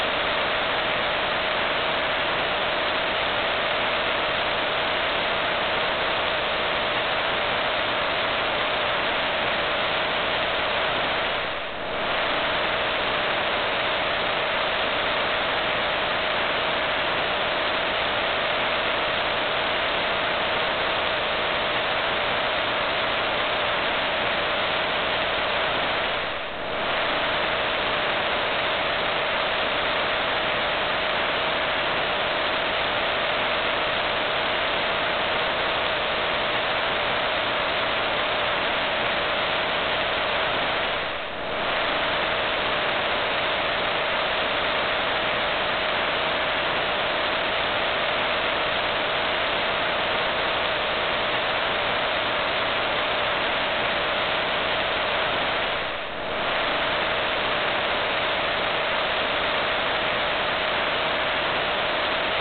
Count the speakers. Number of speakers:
zero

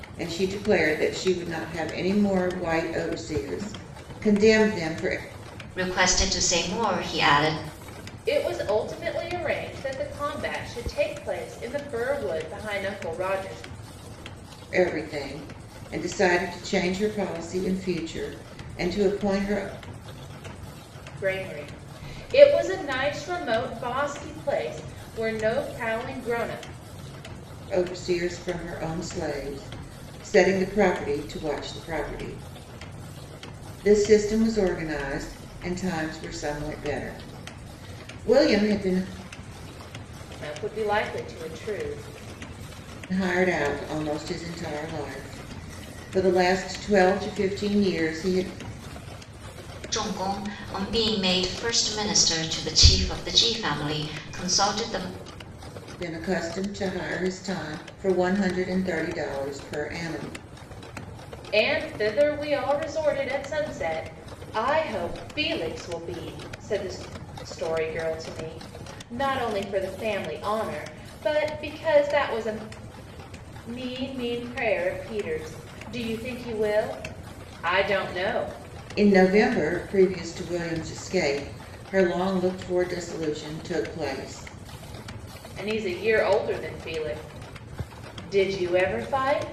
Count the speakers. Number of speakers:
three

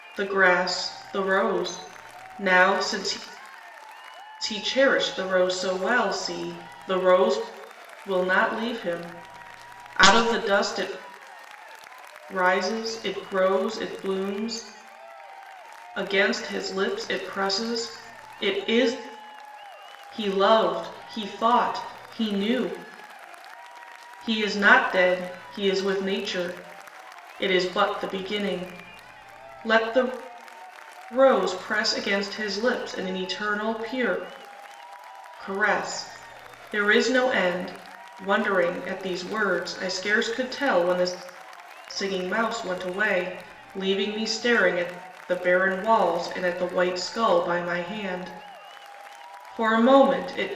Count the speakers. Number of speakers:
one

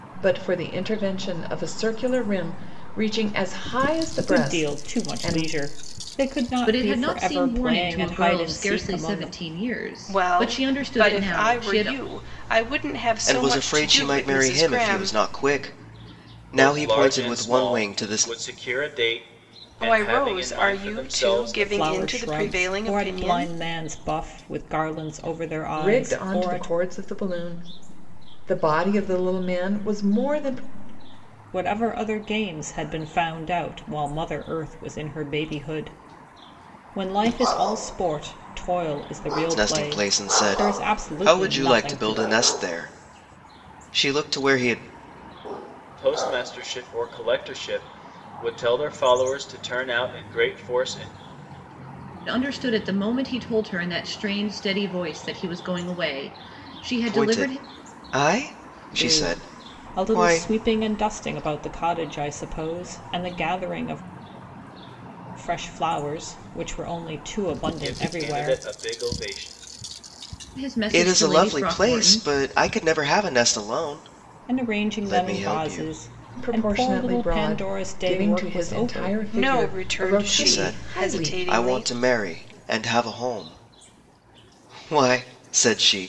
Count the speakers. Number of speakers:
six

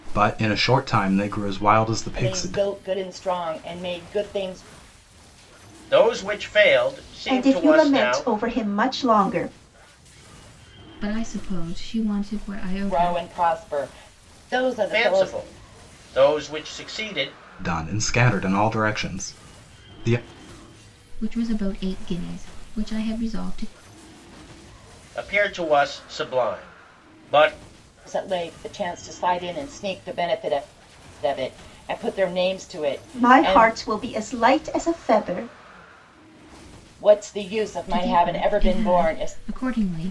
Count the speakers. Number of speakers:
five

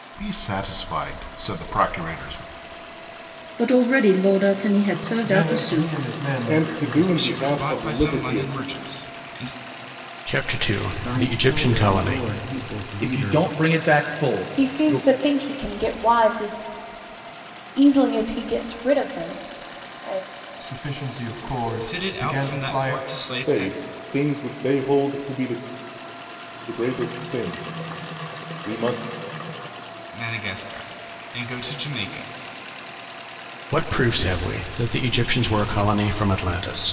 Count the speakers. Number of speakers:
nine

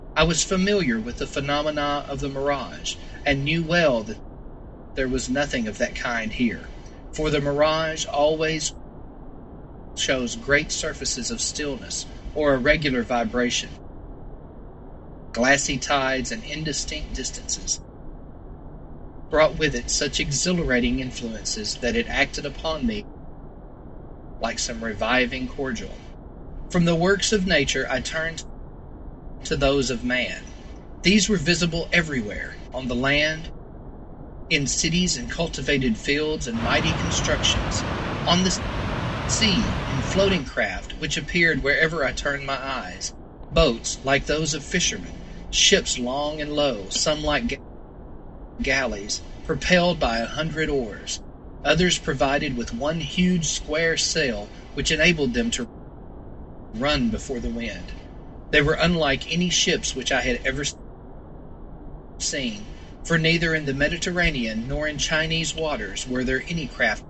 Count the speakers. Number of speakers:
one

